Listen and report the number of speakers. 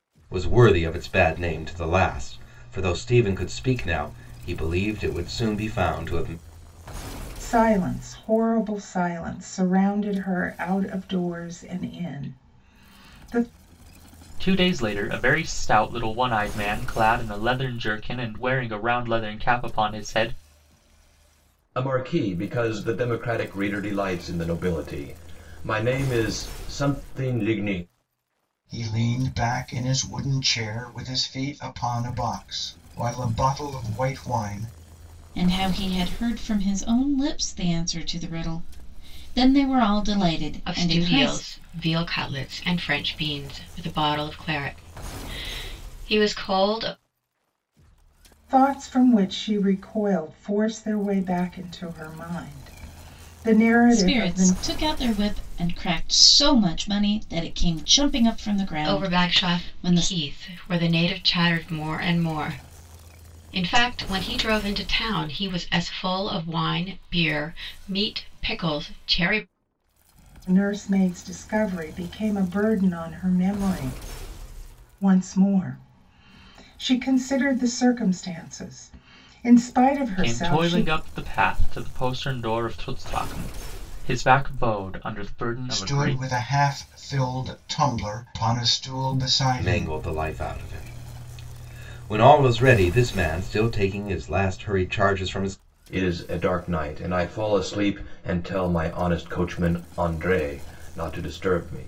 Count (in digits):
7